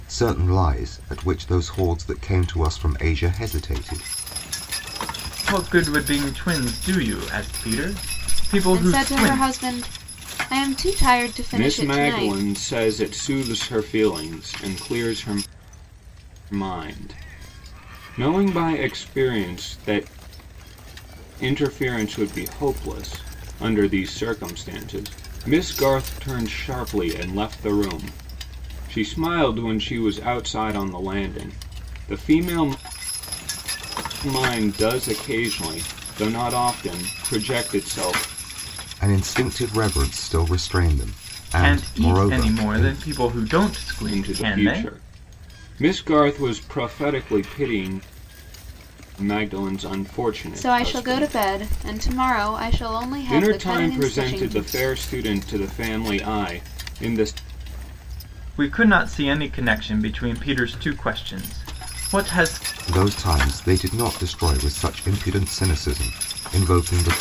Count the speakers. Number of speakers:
four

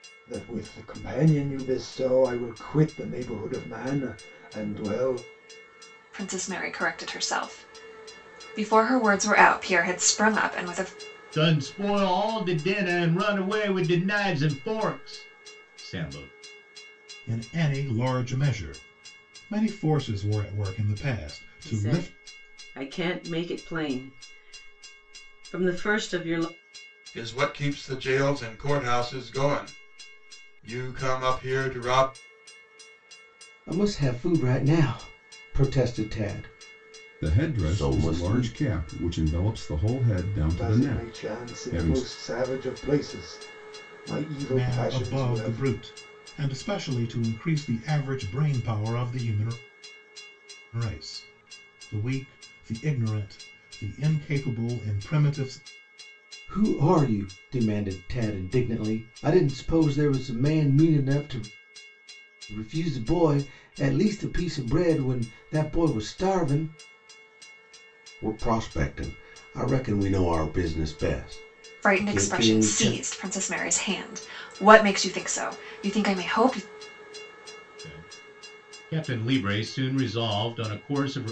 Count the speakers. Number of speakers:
eight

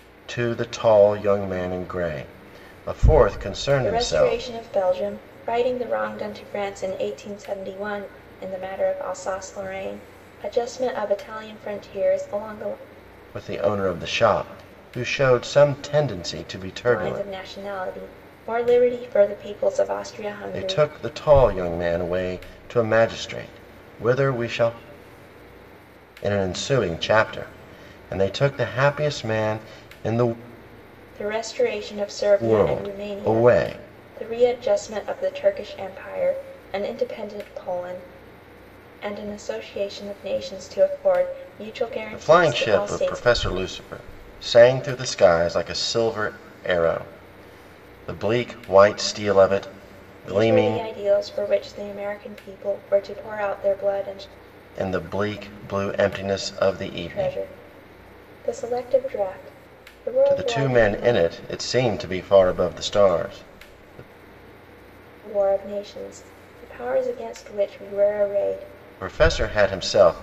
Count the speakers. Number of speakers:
two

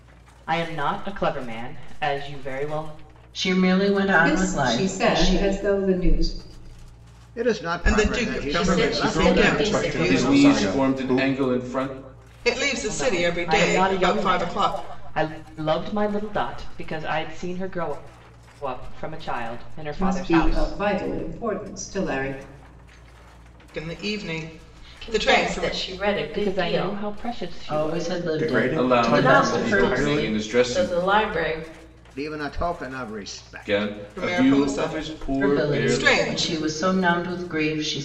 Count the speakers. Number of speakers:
eight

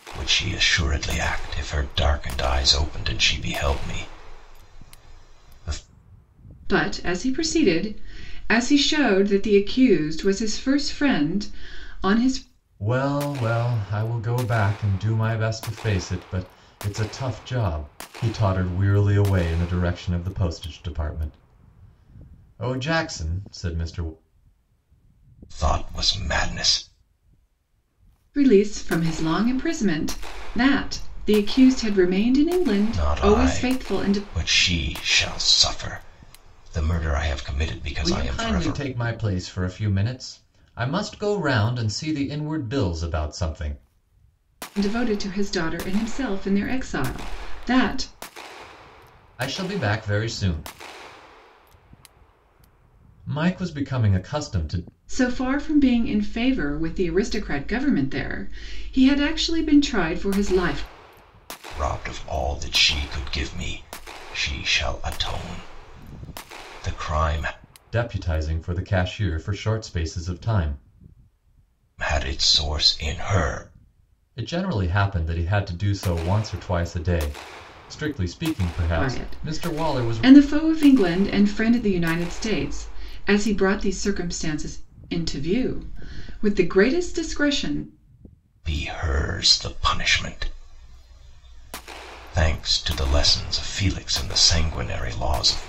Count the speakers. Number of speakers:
three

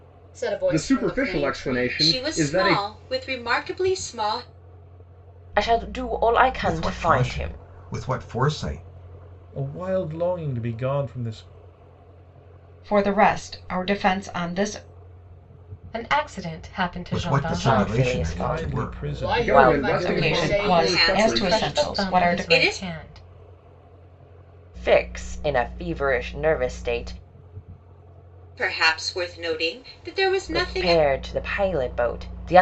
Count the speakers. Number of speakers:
eight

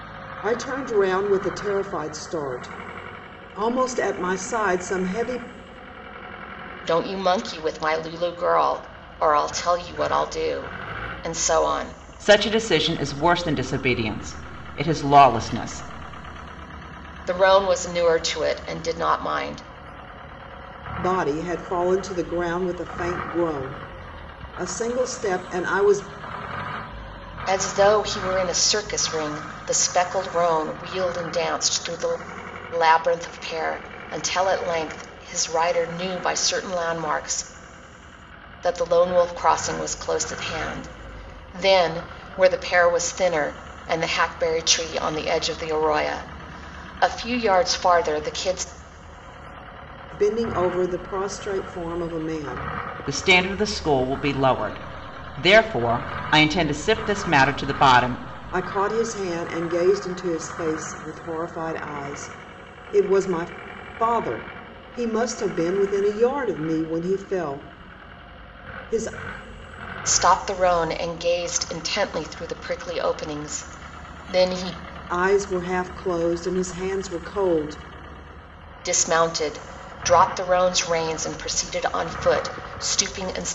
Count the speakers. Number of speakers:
three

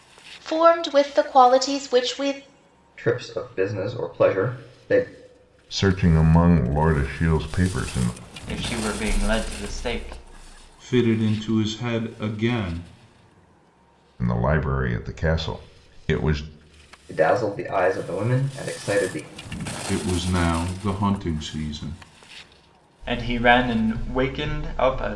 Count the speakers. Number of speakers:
five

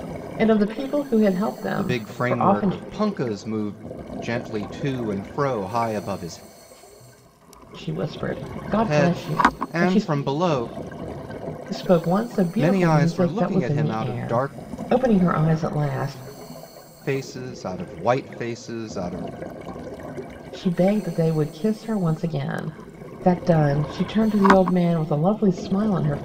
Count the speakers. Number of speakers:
two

